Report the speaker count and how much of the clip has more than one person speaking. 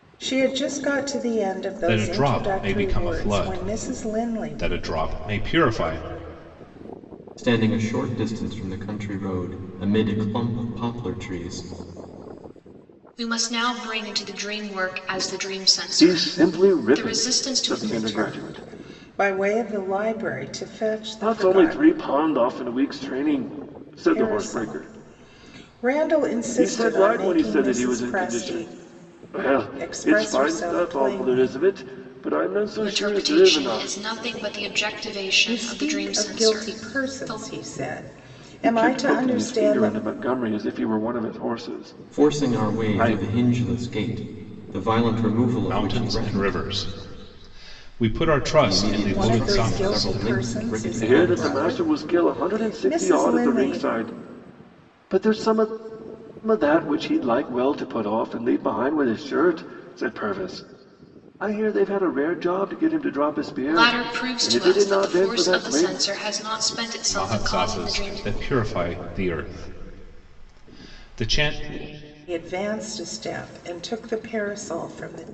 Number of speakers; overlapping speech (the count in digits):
5, about 36%